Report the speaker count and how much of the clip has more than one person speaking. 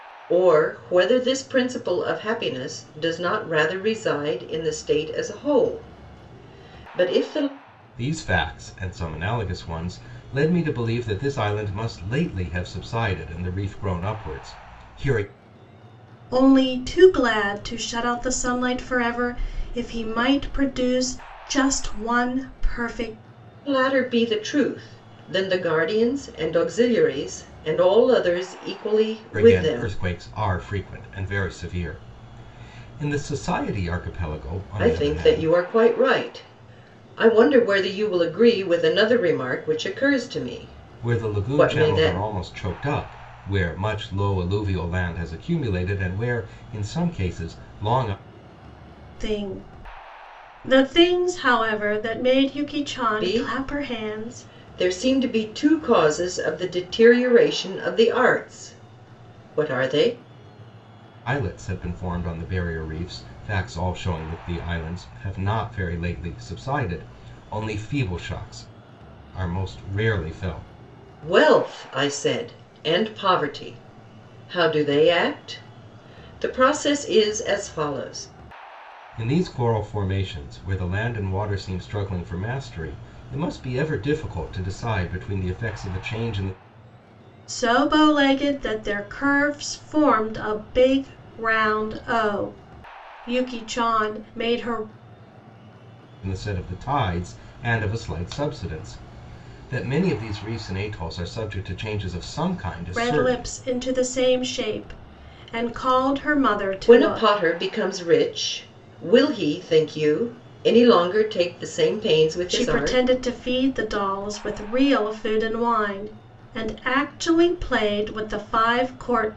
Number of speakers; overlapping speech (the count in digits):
3, about 5%